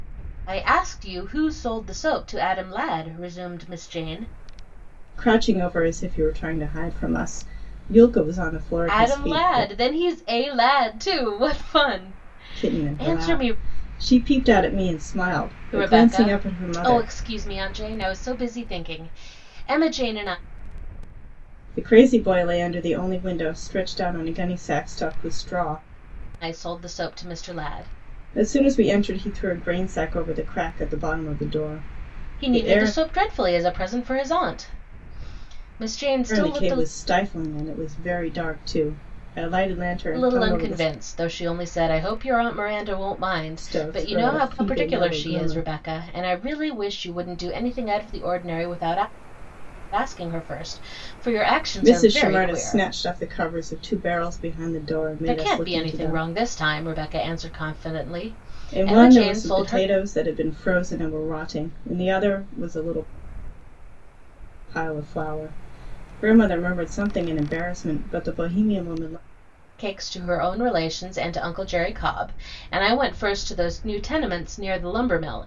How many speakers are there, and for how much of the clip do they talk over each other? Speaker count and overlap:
two, about 14%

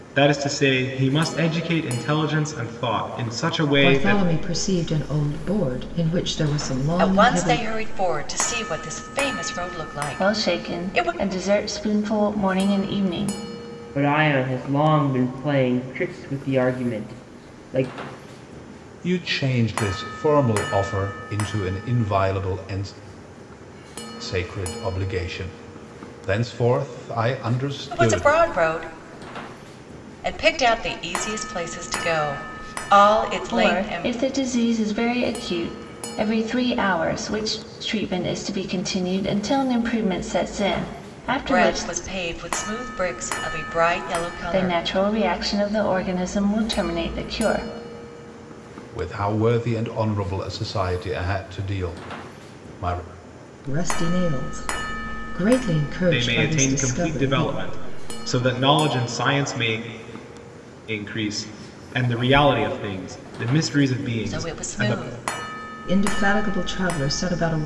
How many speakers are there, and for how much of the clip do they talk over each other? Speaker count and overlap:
six, about 10%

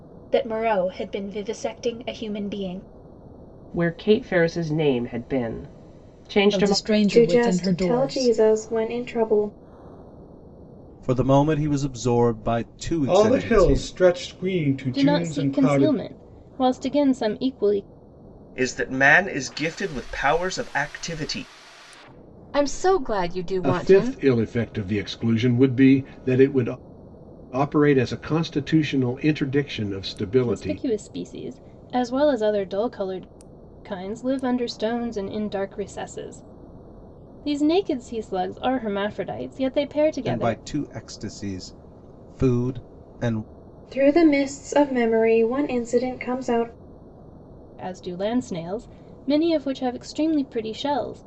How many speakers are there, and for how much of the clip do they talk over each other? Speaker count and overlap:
ten, about 10%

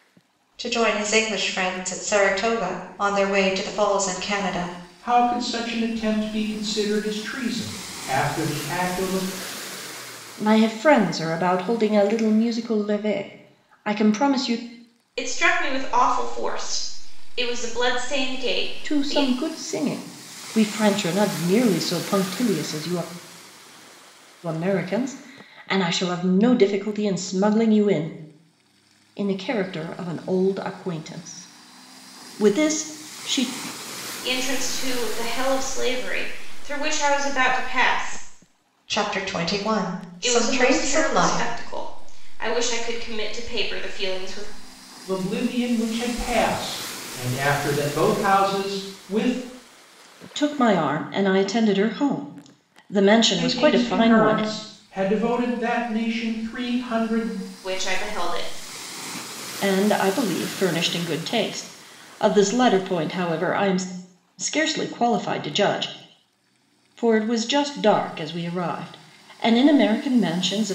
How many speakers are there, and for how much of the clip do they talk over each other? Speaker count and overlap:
four, about 4%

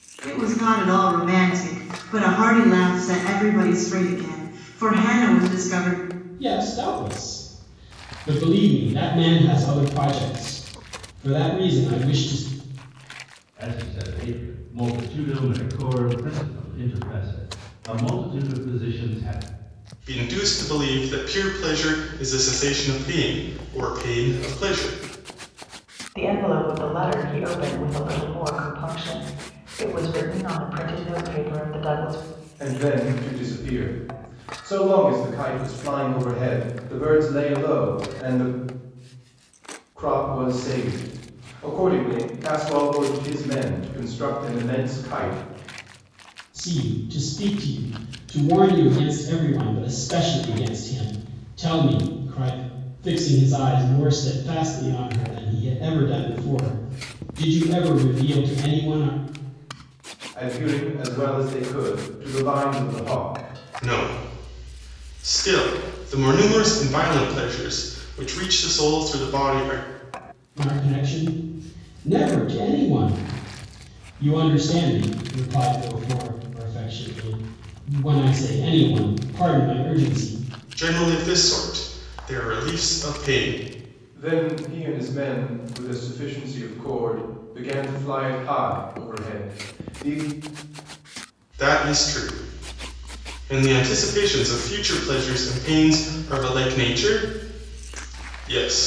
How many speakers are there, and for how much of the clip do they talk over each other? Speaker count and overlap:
six, no overlap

